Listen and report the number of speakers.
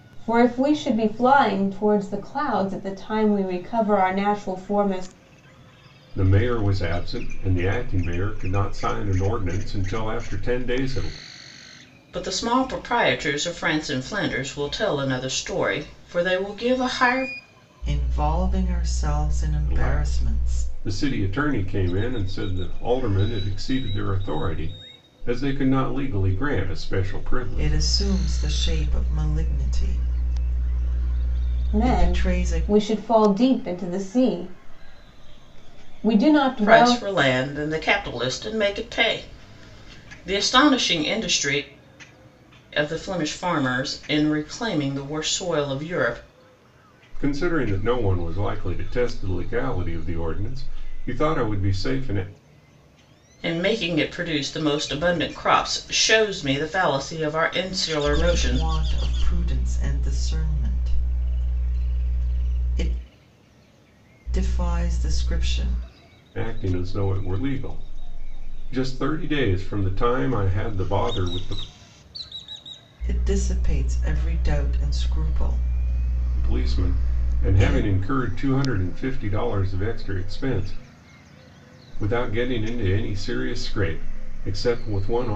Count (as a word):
four